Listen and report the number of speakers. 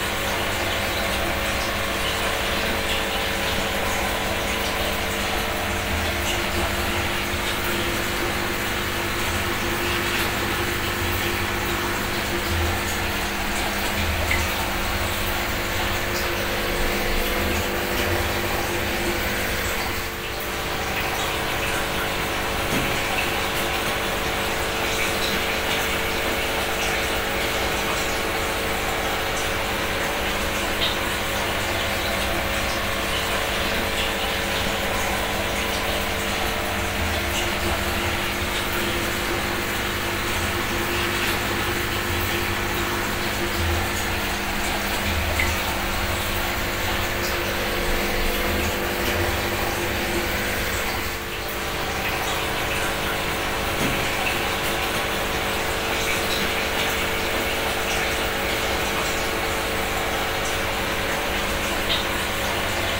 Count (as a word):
zero